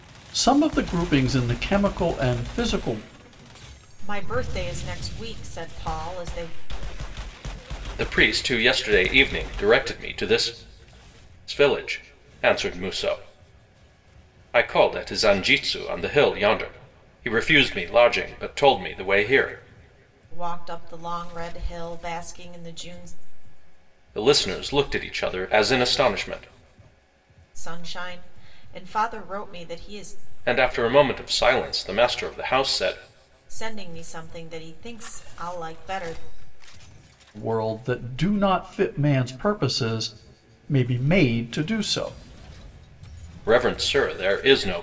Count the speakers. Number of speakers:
three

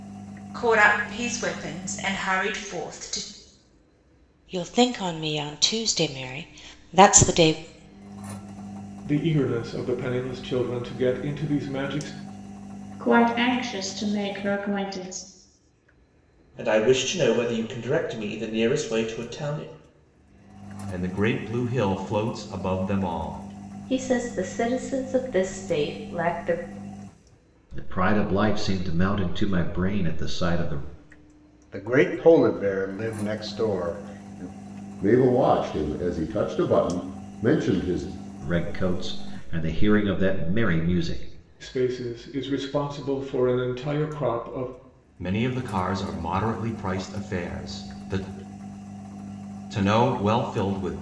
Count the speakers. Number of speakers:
ten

